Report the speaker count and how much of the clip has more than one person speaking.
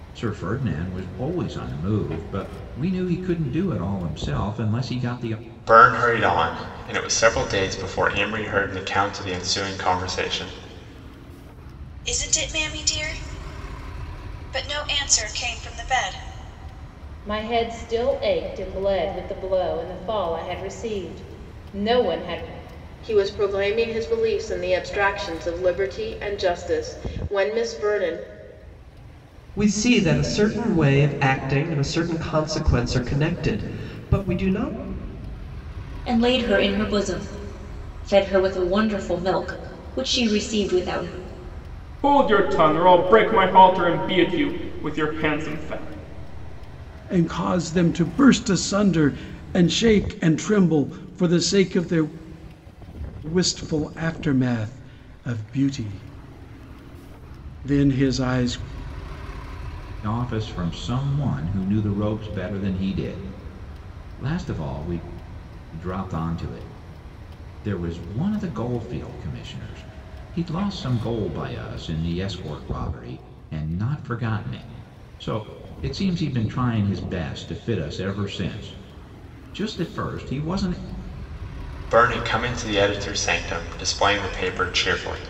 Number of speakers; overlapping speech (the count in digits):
9, no overlap